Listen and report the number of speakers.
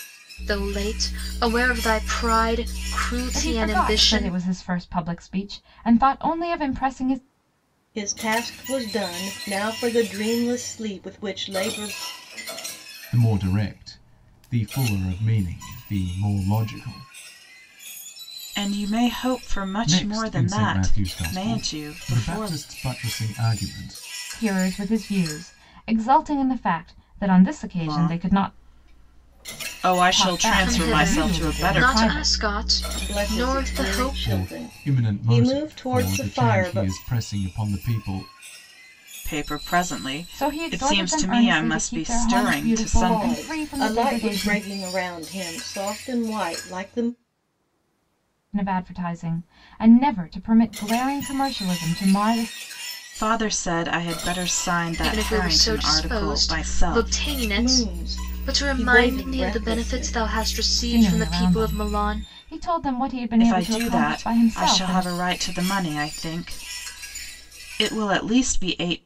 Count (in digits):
5